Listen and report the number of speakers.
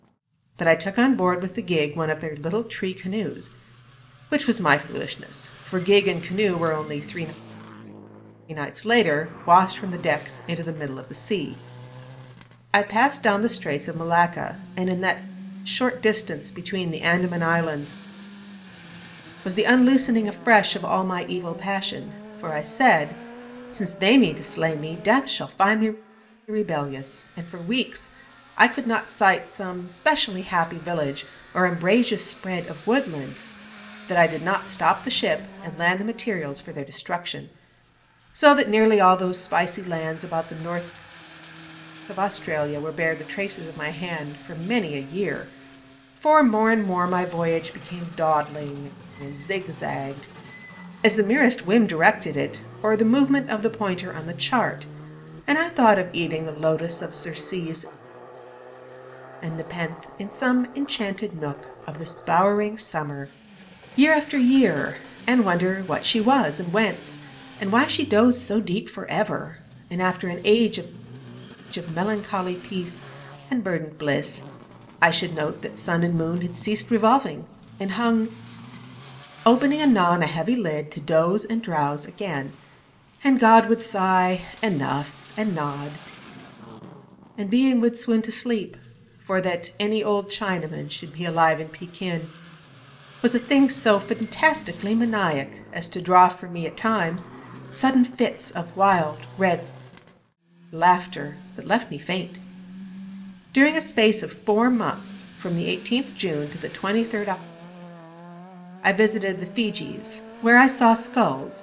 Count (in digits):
1